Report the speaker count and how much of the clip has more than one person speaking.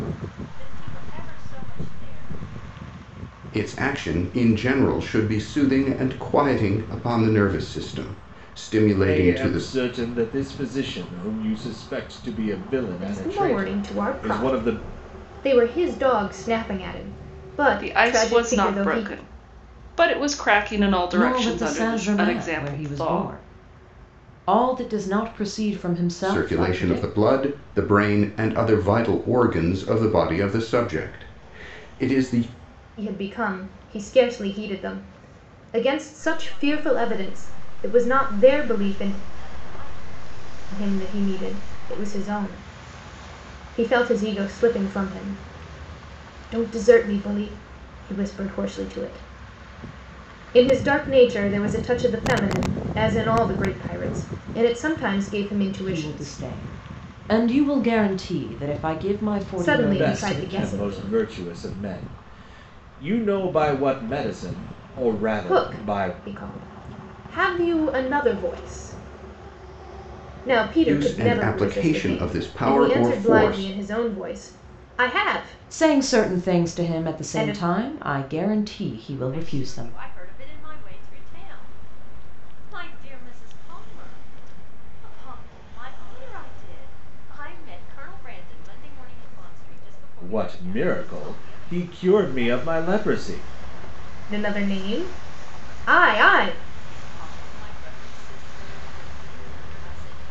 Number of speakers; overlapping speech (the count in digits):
6, about 25%